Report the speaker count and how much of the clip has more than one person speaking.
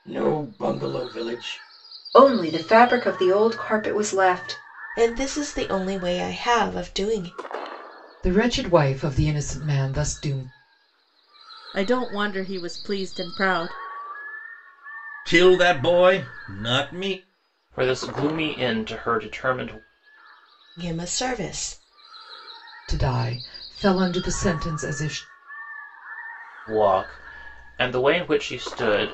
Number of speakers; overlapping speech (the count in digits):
7, no overlap